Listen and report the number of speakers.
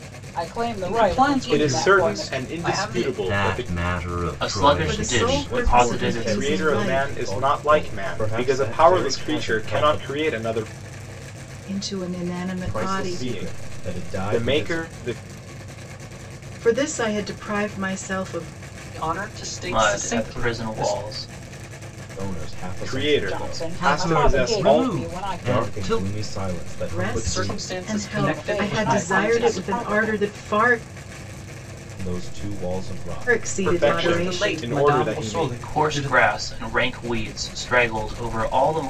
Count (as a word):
seven